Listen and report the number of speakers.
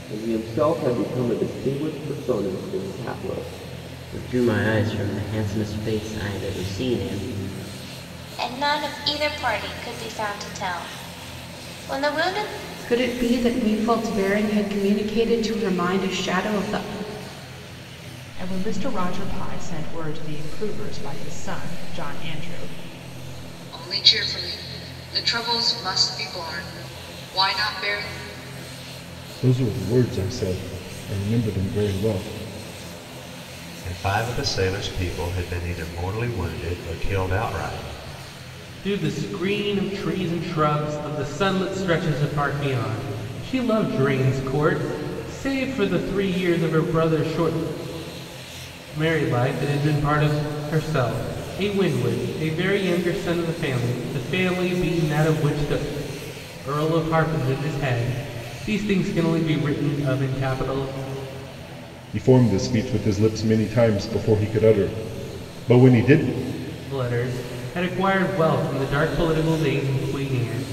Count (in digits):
9